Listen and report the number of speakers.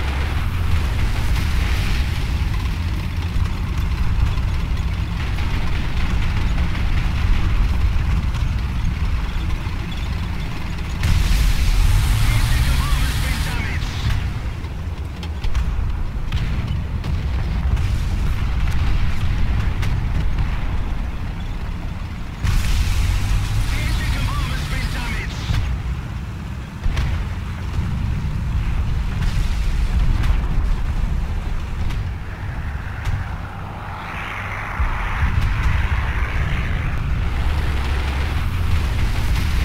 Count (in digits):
0